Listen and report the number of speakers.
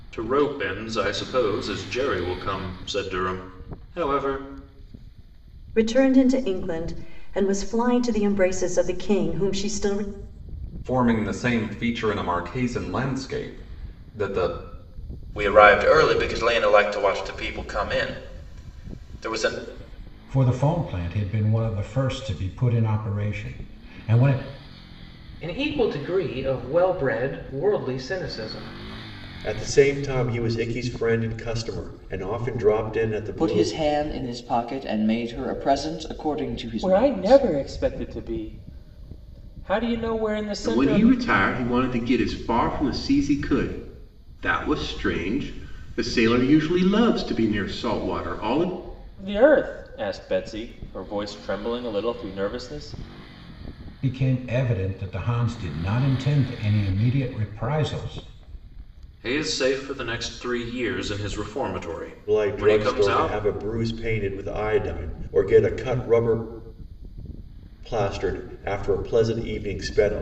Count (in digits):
10